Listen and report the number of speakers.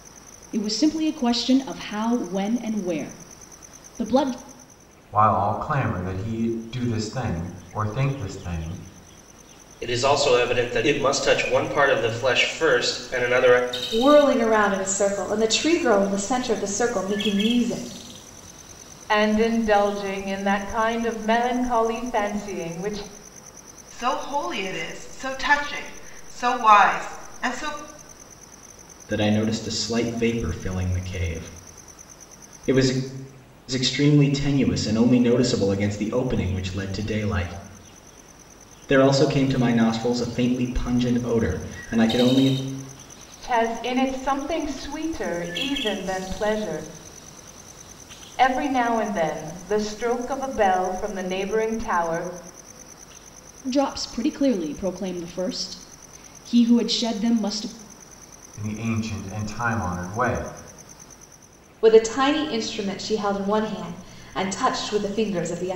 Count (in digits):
7